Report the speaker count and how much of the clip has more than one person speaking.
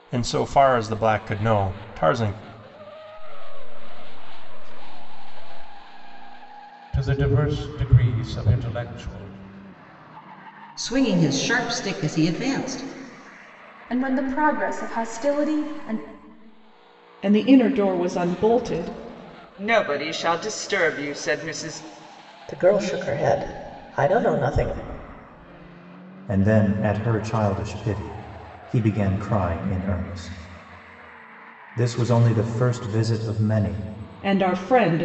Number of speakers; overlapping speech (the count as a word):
nine, no overlap